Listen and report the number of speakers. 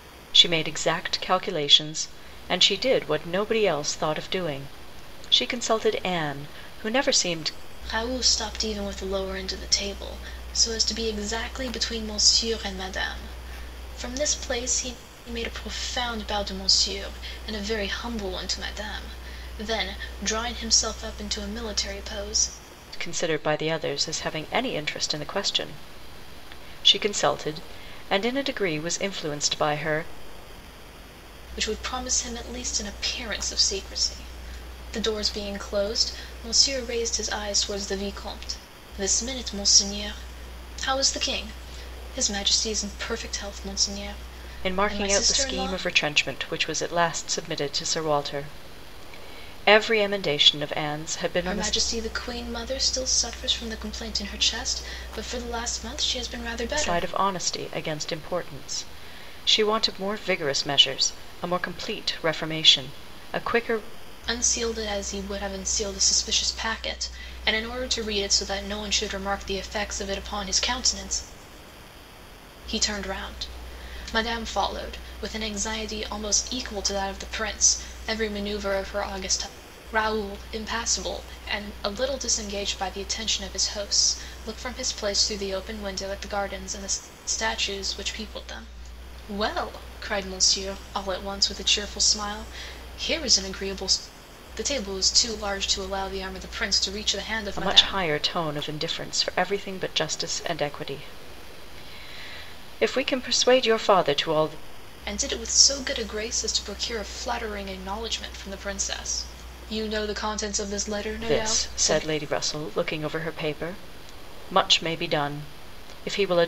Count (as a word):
two